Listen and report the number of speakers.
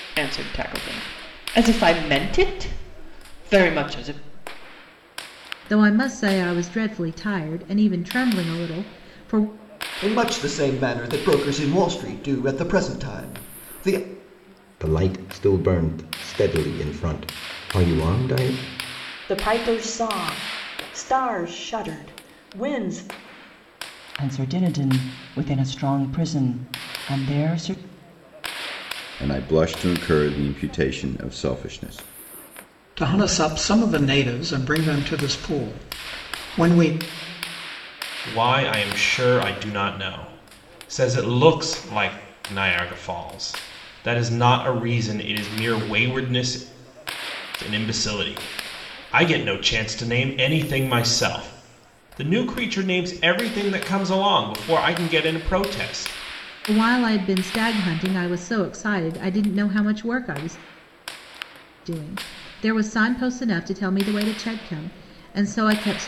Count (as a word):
nine